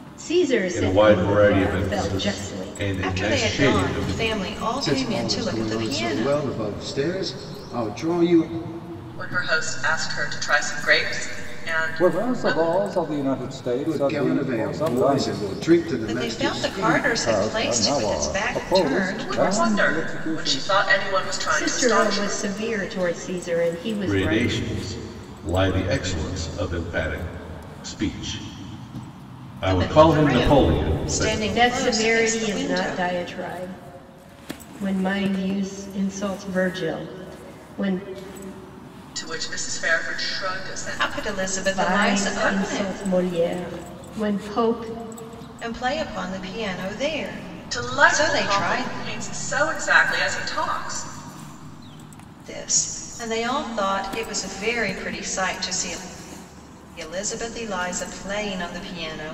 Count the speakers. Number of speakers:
6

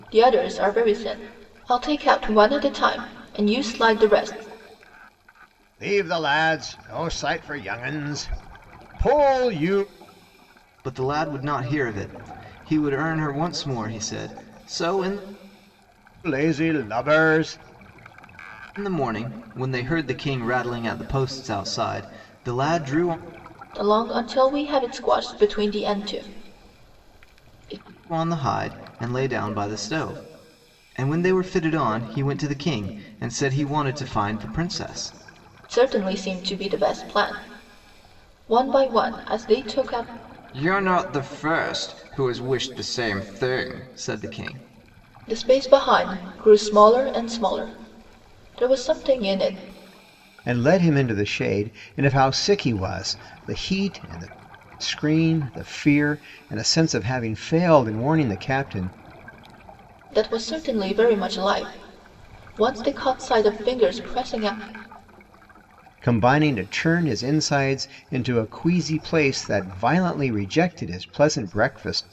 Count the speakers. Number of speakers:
3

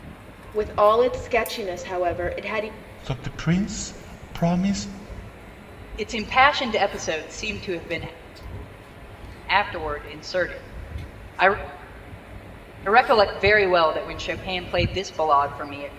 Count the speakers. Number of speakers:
3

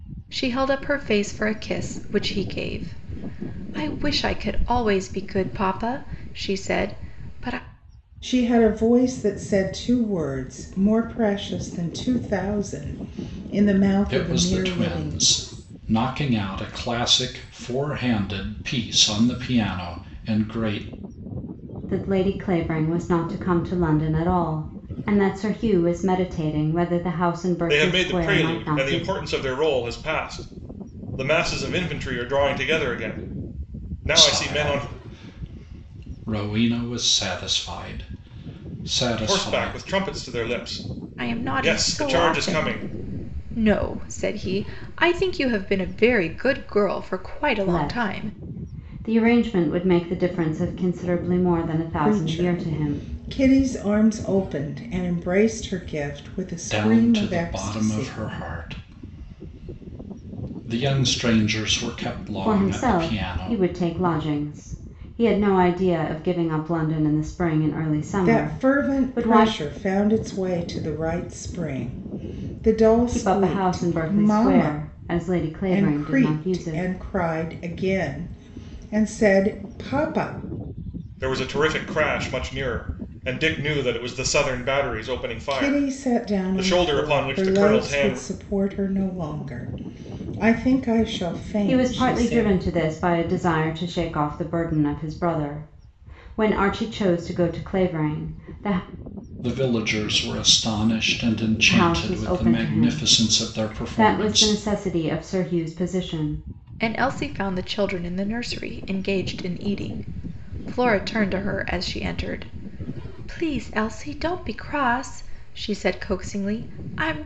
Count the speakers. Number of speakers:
5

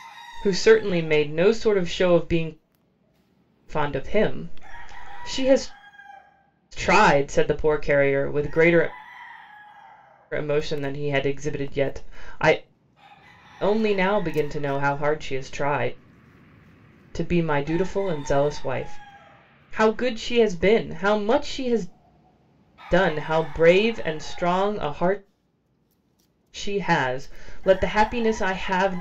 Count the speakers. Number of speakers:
1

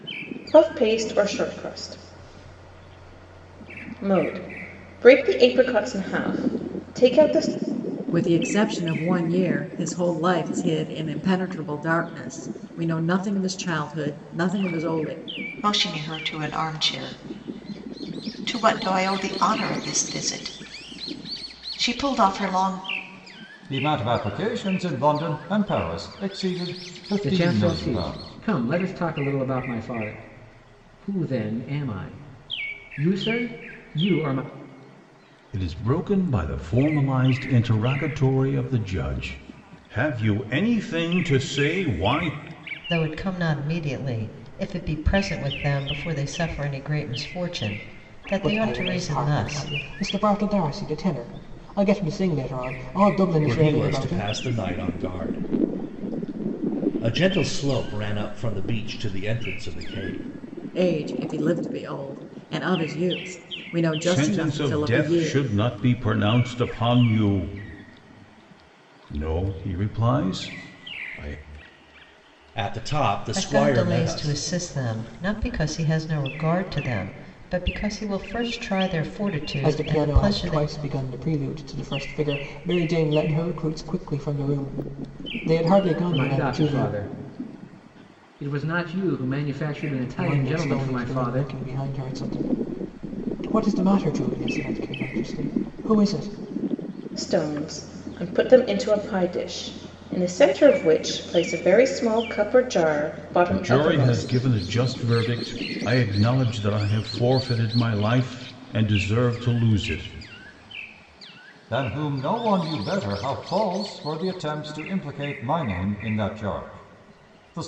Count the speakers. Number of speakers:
9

